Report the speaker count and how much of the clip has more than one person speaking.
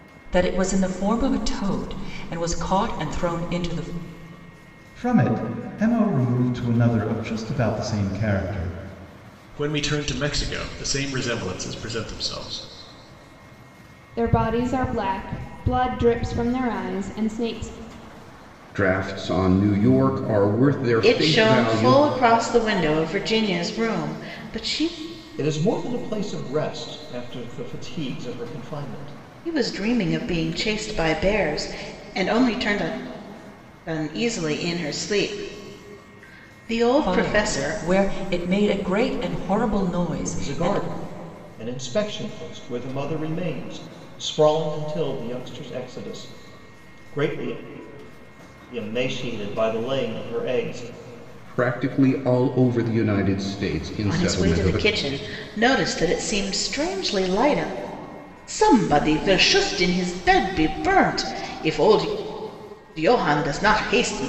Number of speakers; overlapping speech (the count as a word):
seven, about 5%